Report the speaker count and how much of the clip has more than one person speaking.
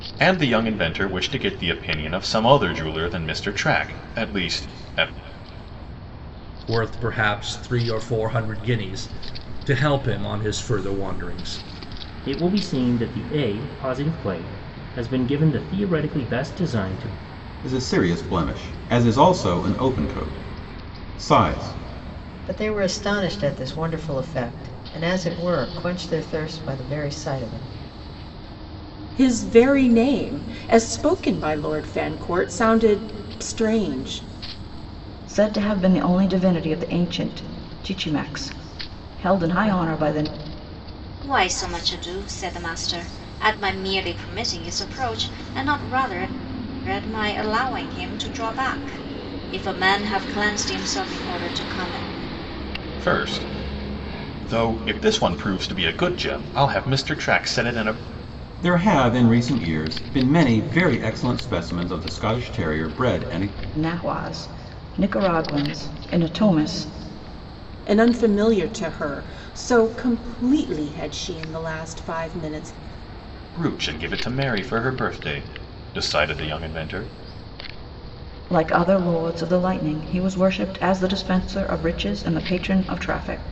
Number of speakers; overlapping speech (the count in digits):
8, no overlap